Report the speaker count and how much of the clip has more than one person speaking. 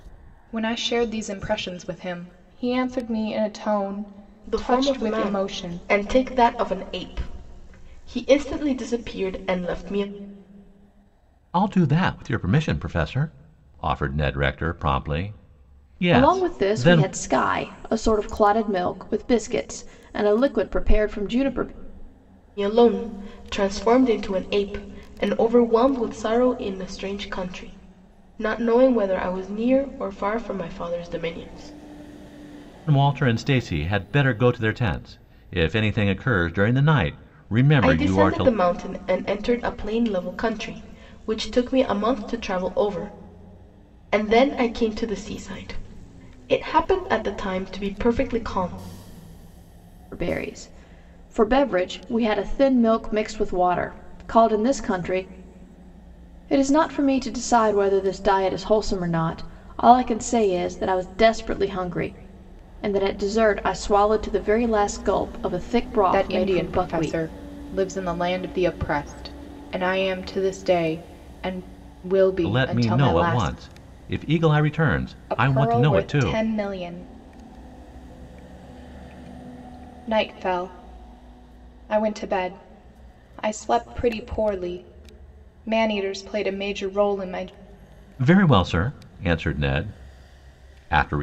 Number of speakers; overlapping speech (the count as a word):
four, about 7%